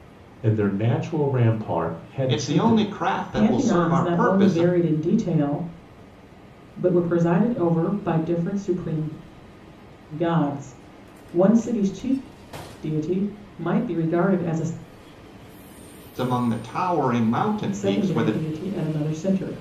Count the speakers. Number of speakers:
three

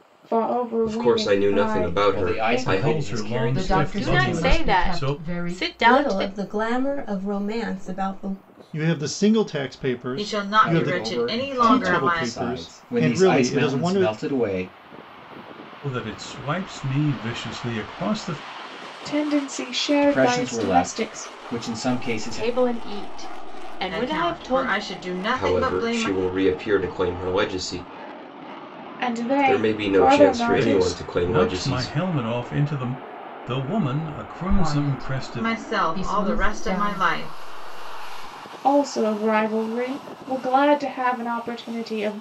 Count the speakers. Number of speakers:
ten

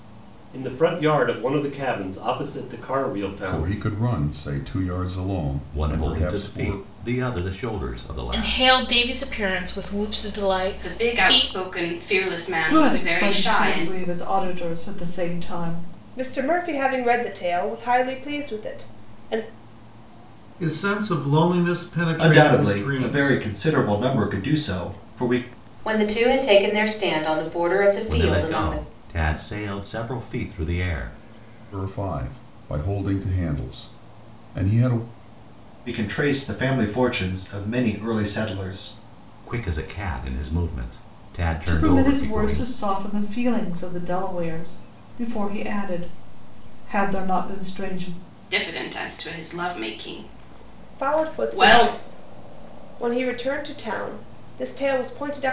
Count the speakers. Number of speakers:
ten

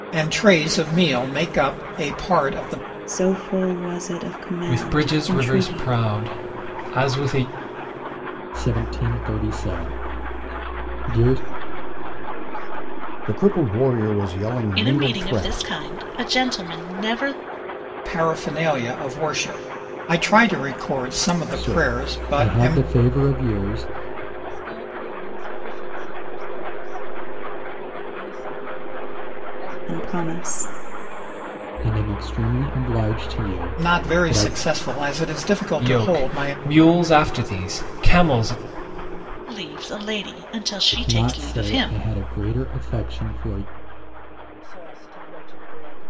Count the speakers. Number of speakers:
seven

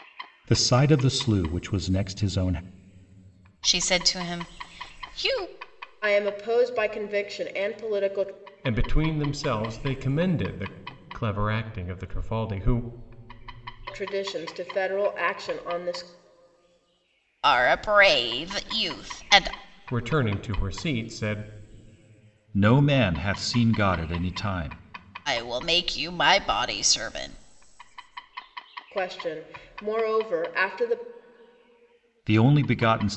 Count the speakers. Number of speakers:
four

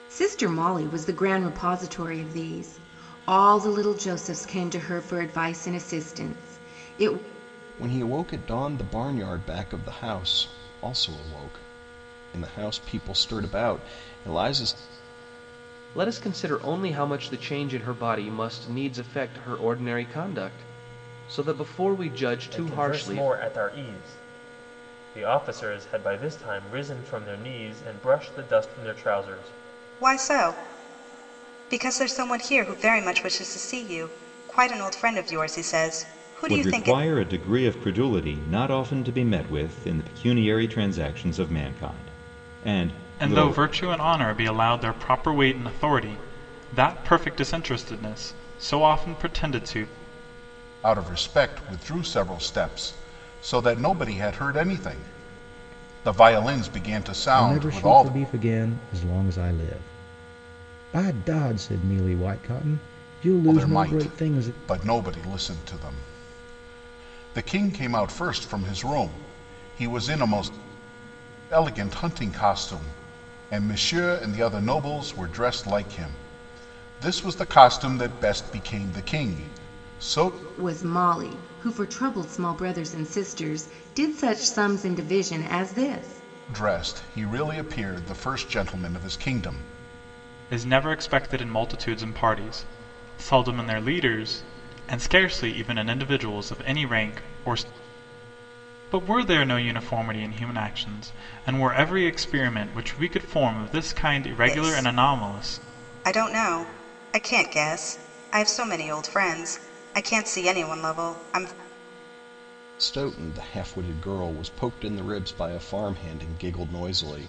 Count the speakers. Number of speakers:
nine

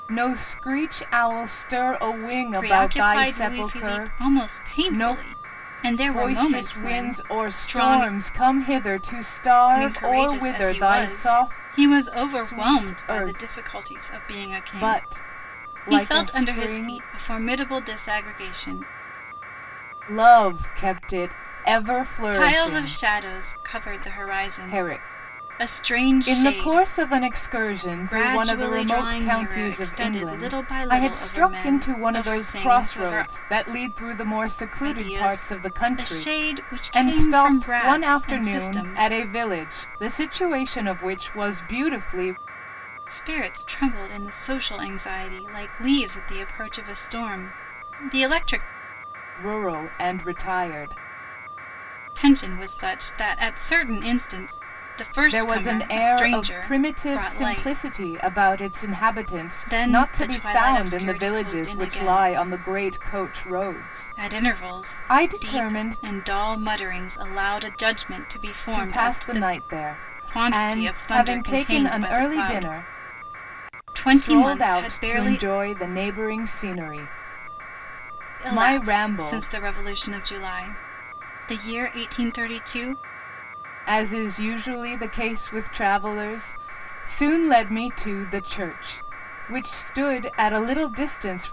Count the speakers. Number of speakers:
two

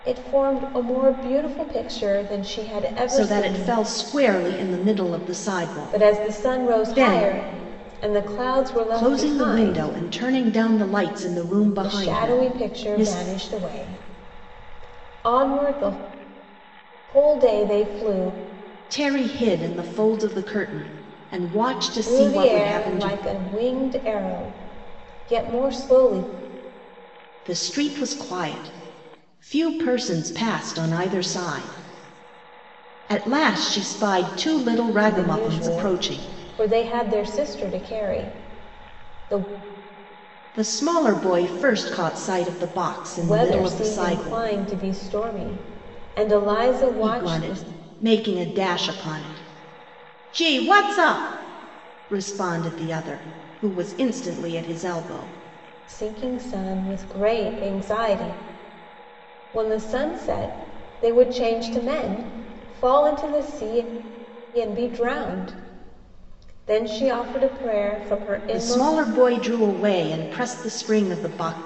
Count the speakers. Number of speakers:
two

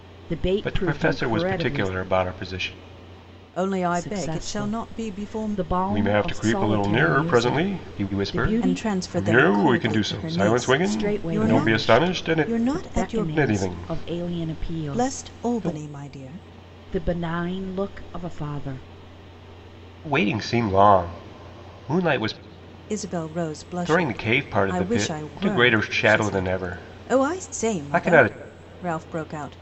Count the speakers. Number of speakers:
three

